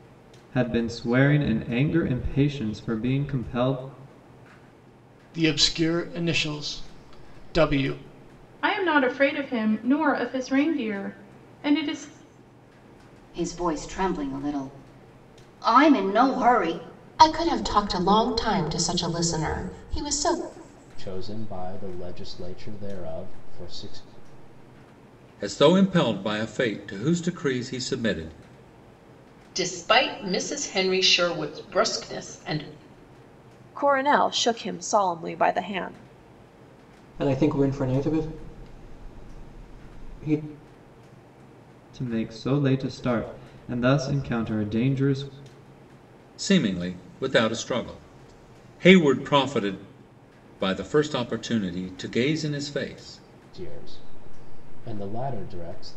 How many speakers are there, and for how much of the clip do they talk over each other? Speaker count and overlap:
ten, no overlap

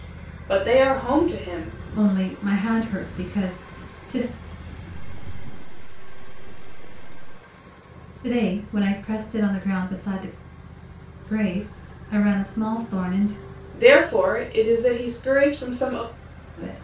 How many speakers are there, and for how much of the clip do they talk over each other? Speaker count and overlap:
three, no overlap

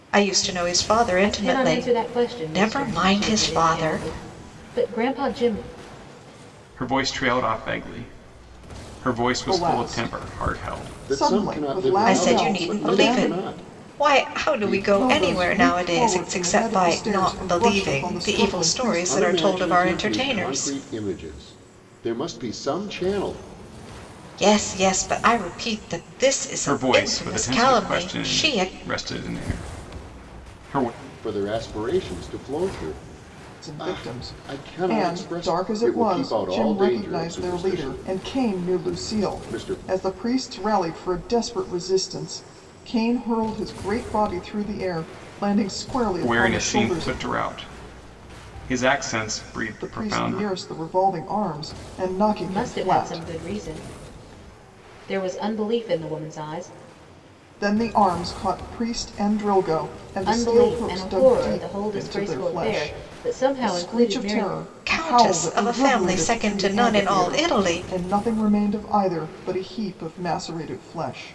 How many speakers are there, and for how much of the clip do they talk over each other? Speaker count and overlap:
five, about 44%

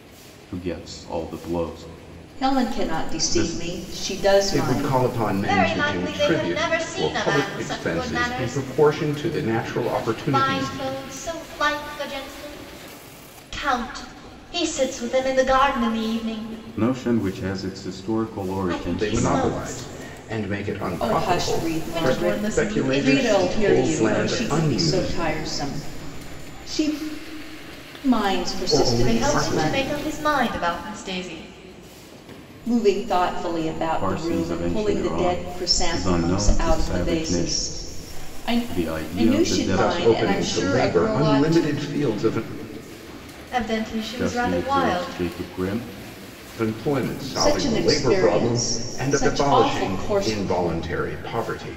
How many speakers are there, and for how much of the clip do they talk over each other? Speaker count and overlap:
four, about 47%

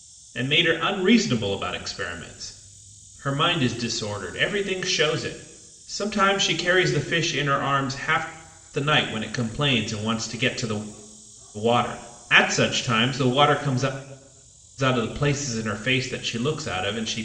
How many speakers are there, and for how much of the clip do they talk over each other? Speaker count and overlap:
one, no overlap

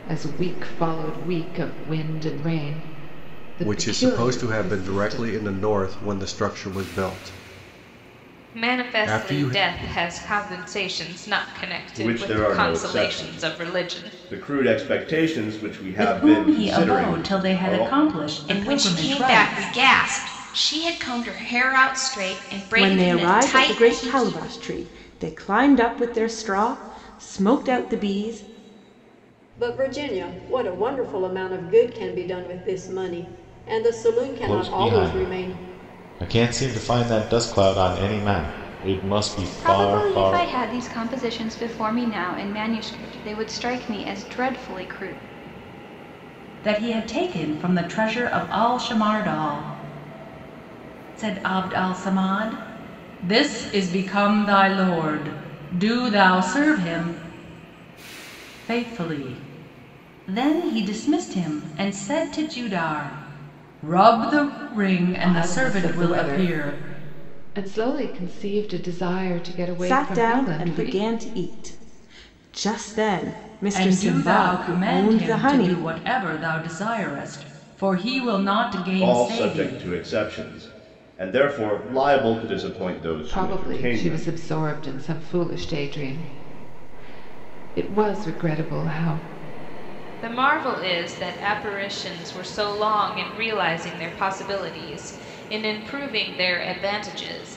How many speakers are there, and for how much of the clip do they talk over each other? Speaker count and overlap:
ten, about 19%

